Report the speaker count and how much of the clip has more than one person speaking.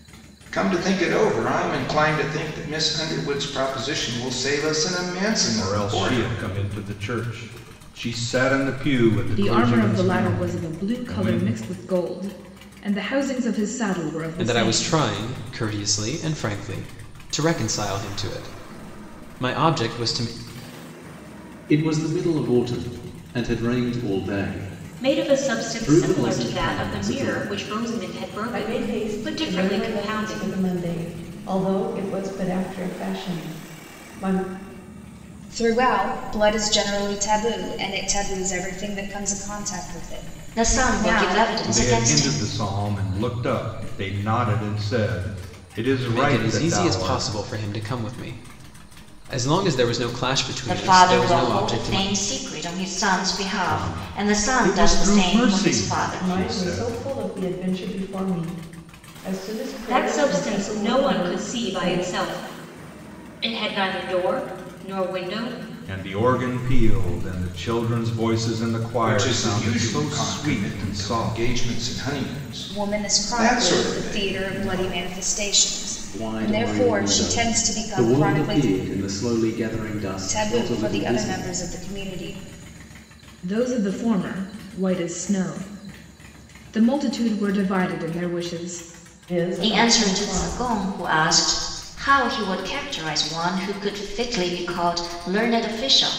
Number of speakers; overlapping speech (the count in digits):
9, about 29%